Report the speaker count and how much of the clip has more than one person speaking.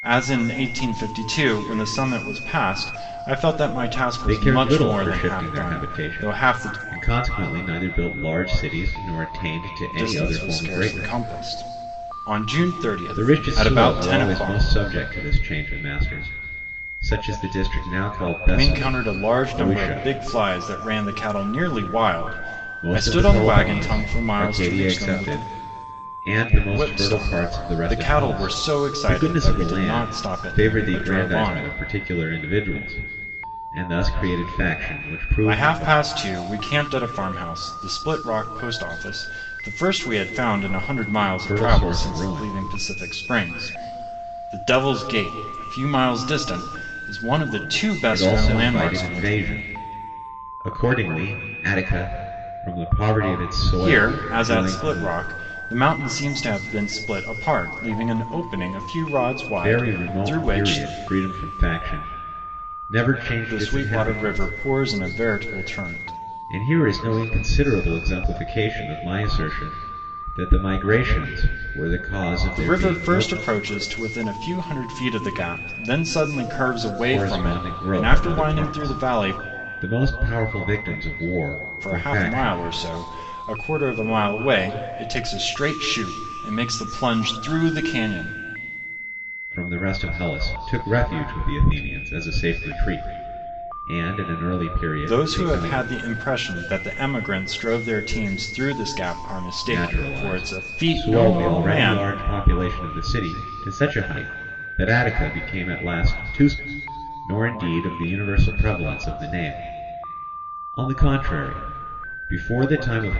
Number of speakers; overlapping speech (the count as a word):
two, about 25%